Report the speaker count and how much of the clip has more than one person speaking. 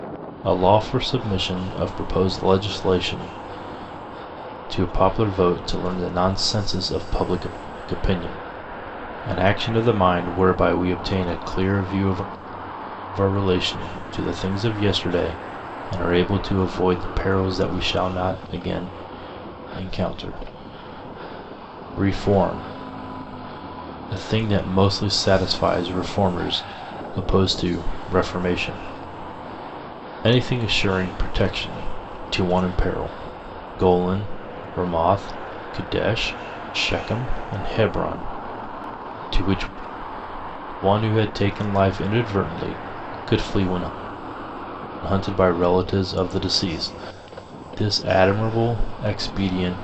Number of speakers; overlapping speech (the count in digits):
1, no overlap